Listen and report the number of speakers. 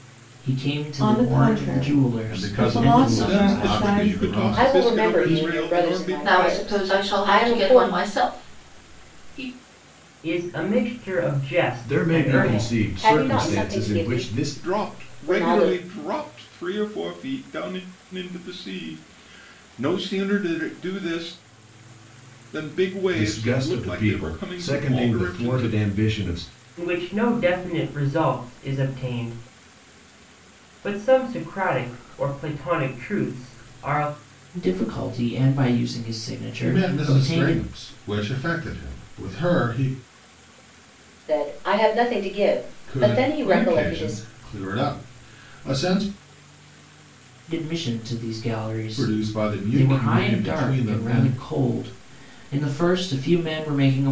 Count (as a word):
eight